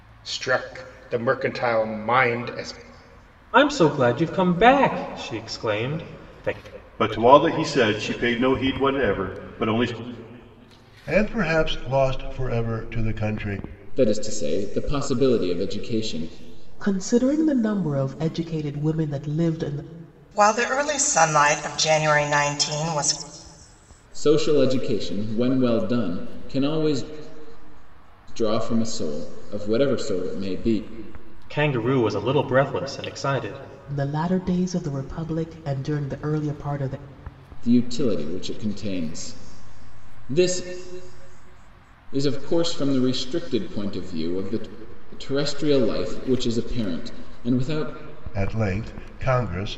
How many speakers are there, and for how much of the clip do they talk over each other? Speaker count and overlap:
7, no overlap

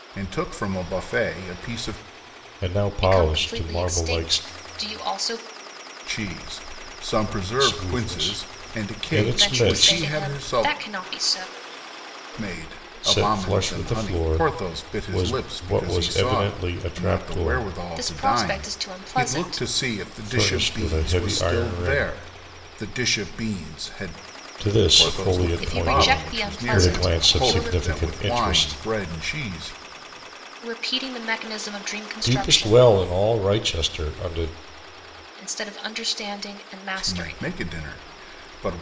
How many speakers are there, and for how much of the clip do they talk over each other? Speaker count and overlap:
3, about 44%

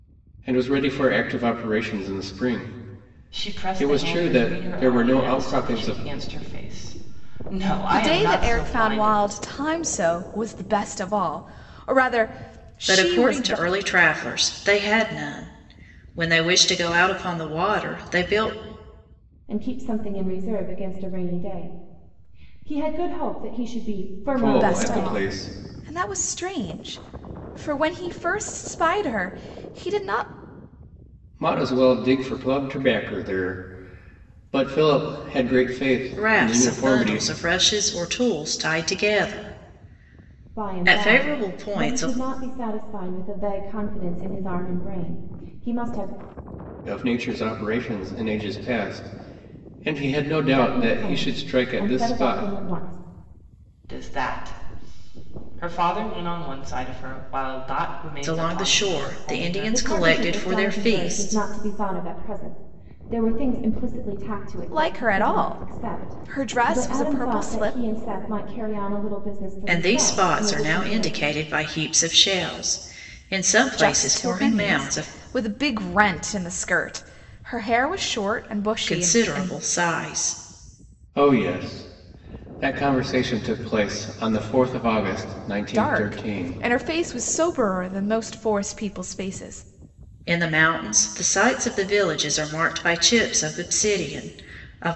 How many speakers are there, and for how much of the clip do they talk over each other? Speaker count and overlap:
5, about 23%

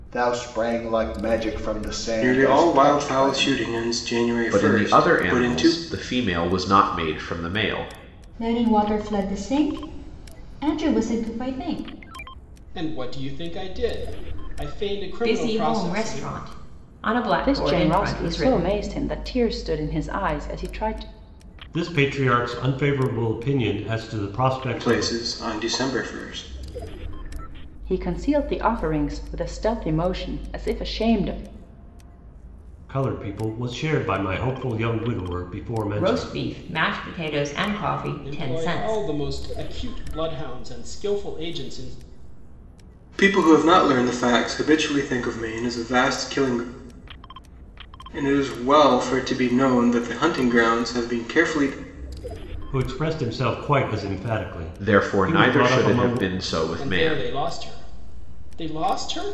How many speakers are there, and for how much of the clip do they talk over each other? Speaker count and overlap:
8, about 15%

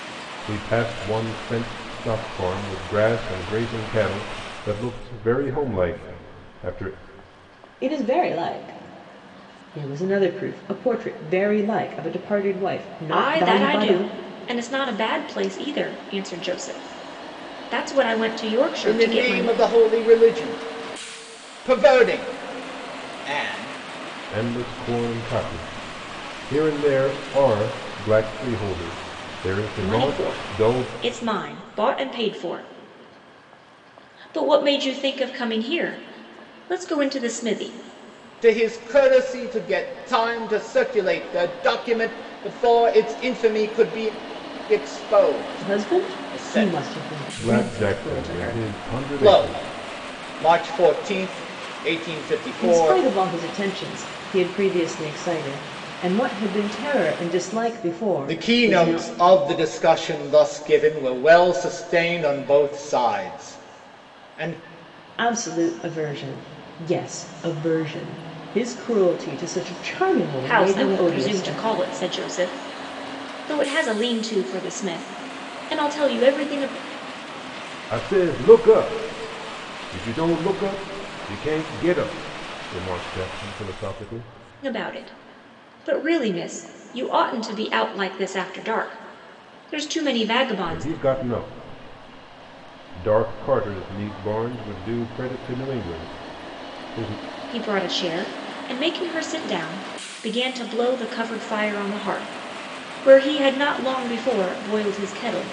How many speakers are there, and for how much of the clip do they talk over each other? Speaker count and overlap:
4, about 8%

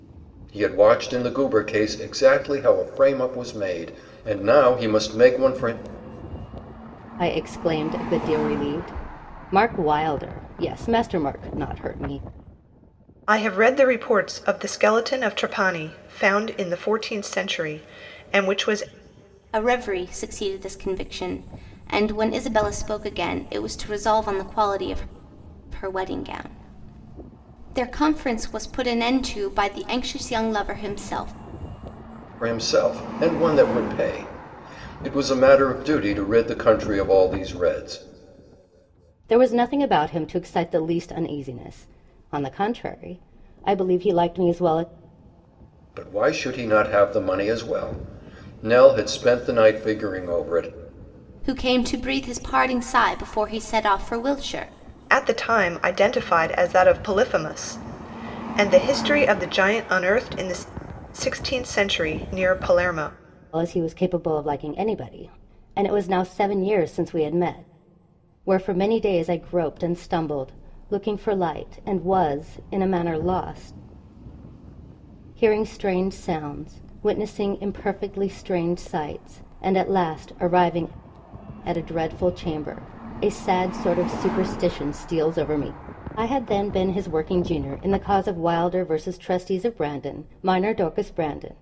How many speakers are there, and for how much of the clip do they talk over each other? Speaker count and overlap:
4, no overlap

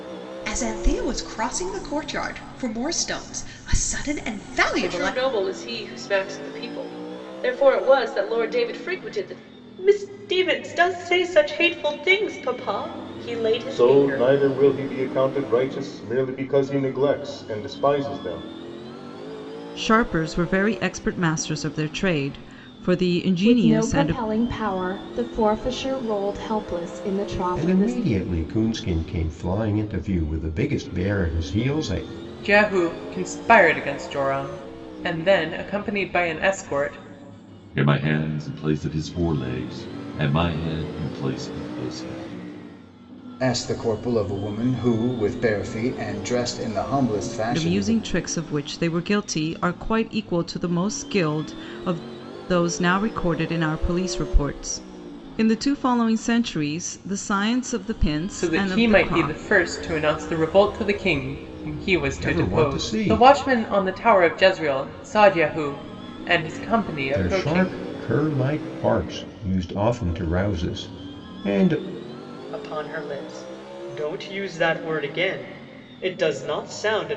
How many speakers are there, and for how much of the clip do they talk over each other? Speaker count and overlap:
10, about 7%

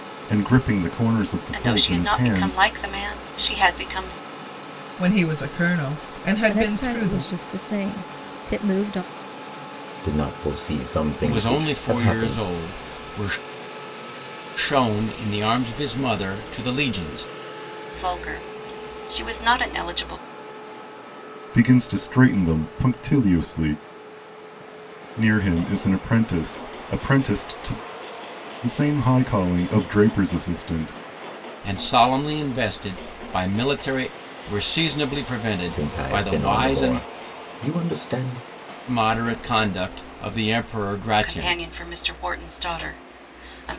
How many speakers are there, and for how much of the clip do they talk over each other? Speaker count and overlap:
6, about 12%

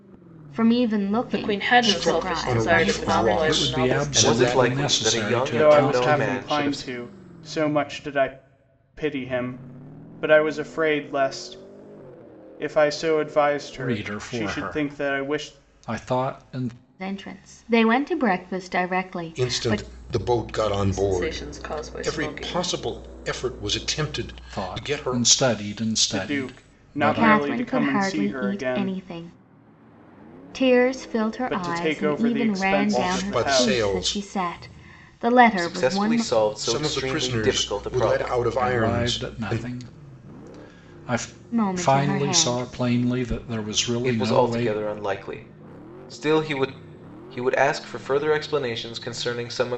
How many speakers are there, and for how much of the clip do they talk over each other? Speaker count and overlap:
6, about 43%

